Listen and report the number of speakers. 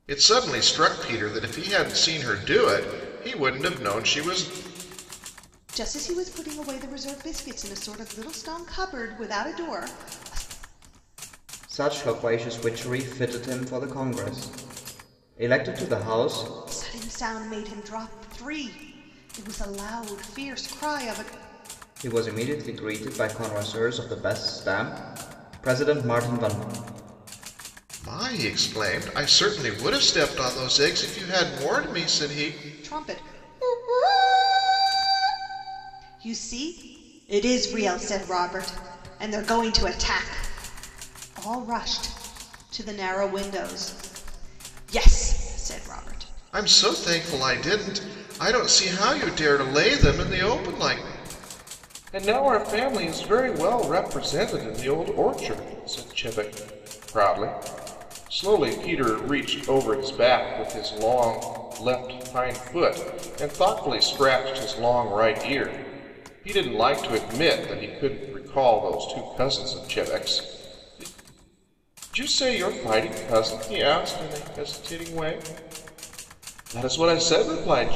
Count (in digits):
3